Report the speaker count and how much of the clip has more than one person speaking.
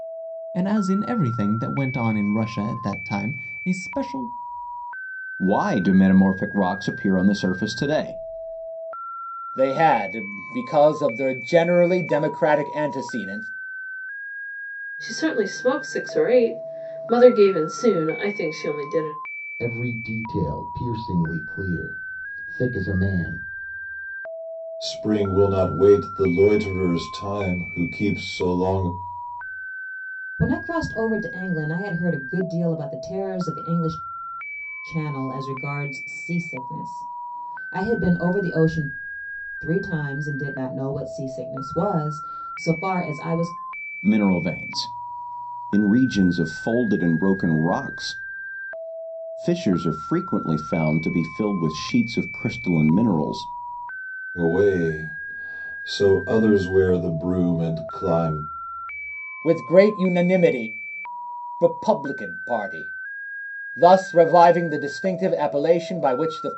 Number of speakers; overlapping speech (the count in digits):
7, no overlap